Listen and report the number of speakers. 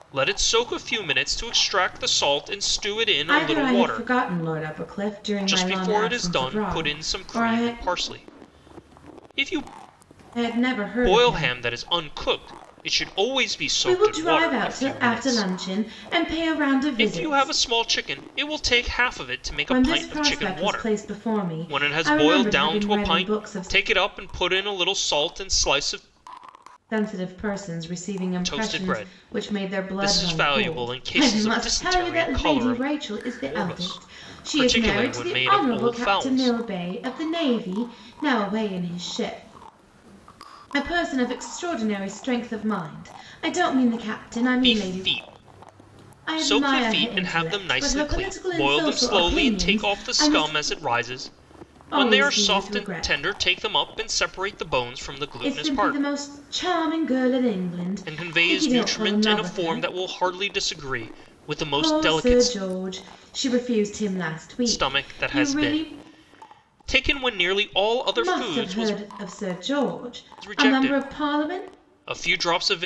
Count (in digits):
2